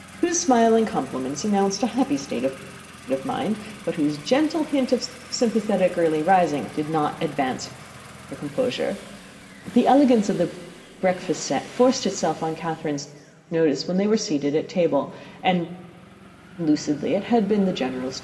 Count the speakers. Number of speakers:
1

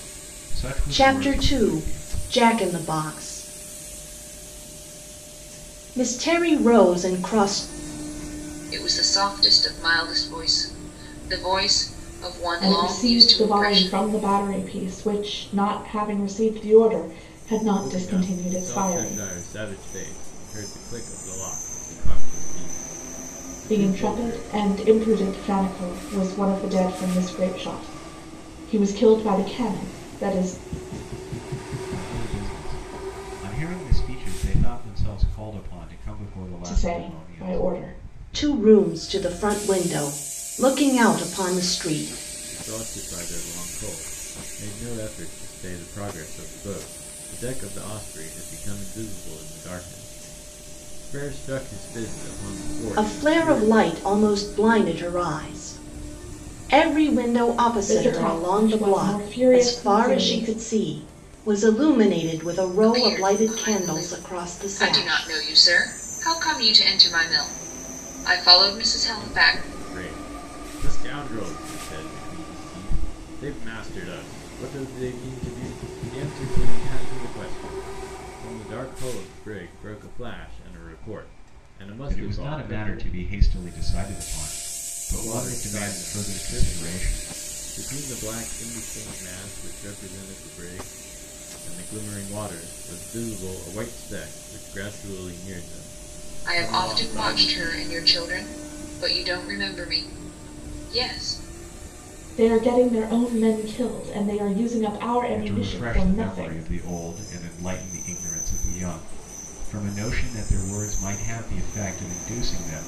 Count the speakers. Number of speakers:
5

